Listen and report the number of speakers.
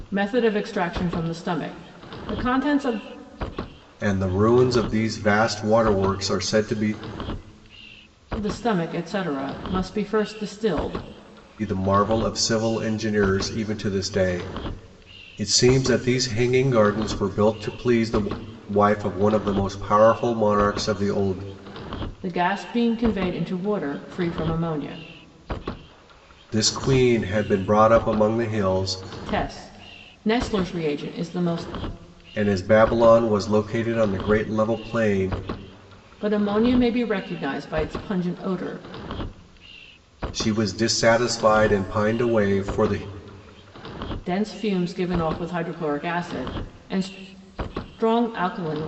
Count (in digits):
2